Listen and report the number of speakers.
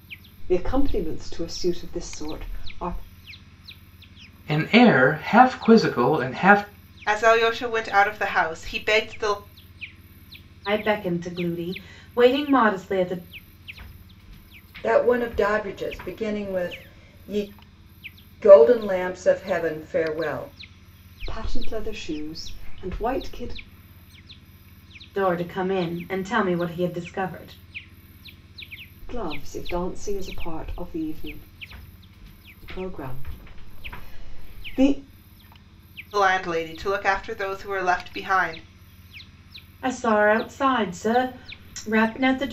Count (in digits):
5